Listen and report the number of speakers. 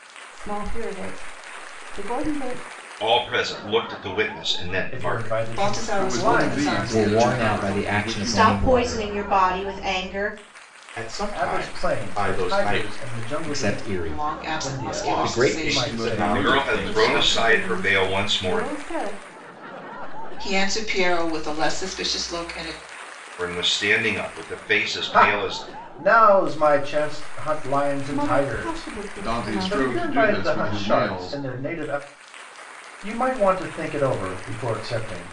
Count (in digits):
9